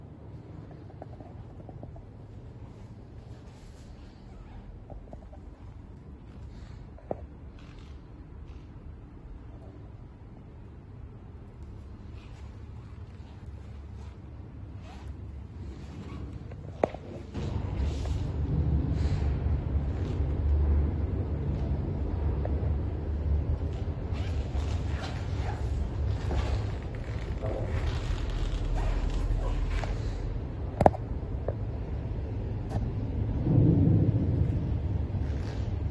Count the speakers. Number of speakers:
zero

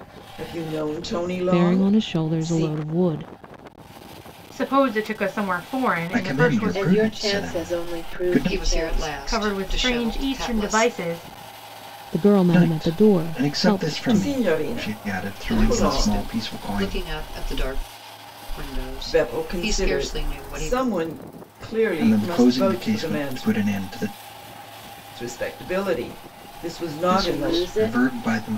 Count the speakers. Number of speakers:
six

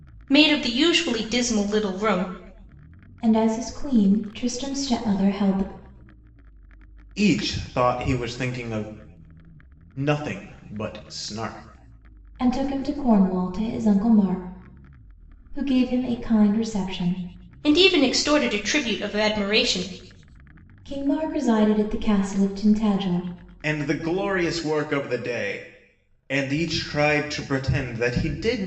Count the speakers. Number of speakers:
three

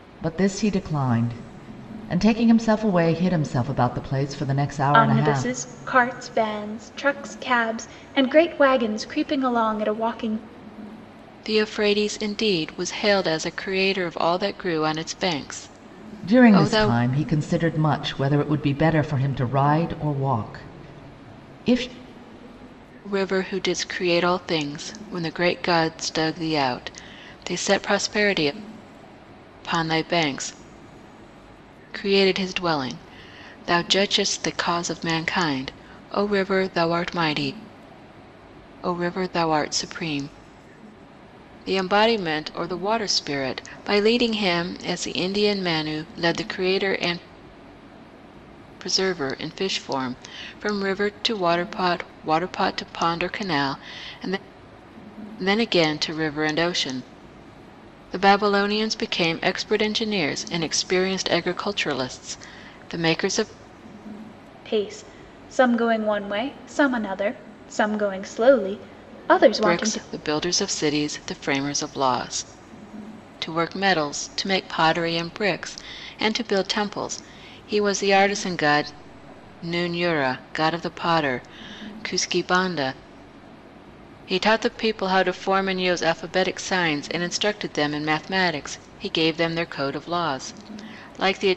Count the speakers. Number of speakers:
three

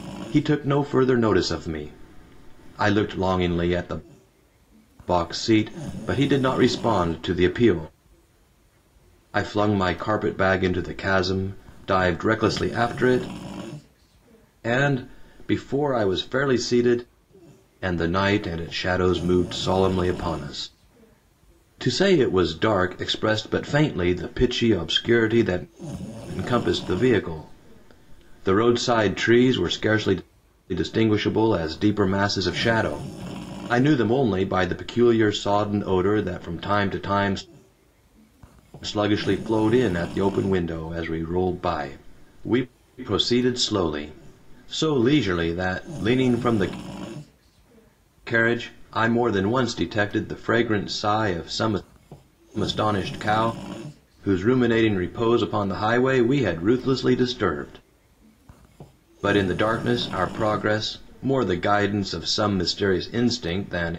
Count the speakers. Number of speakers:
one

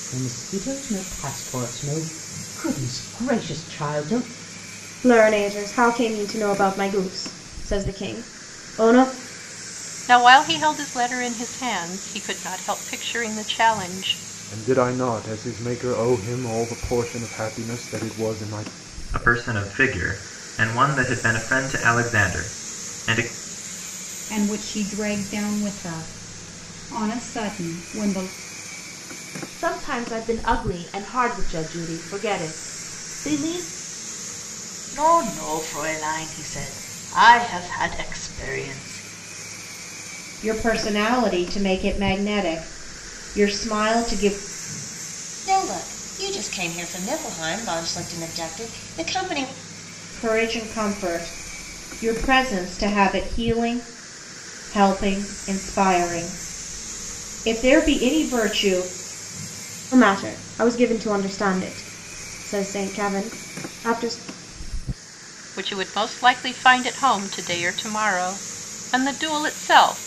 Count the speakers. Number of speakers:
ten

